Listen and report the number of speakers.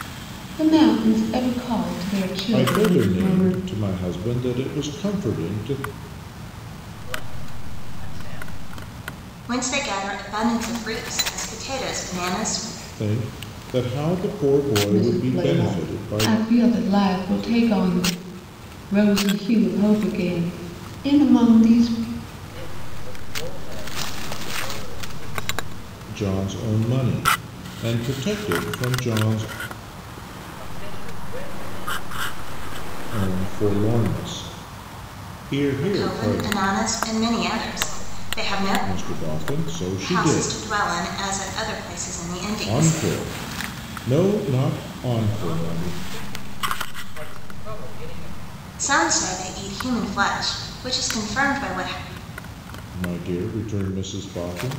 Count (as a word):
four